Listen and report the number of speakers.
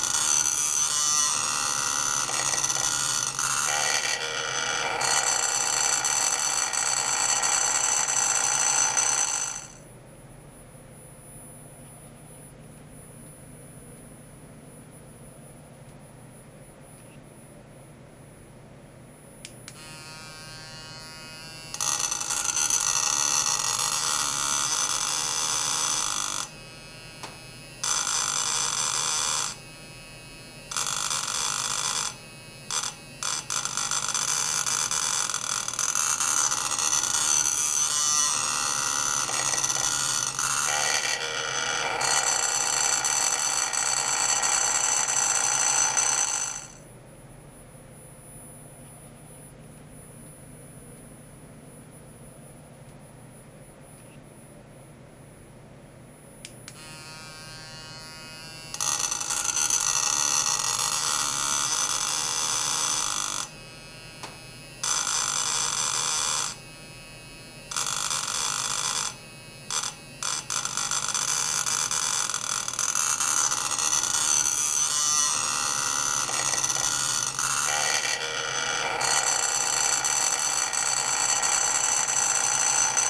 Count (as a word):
zero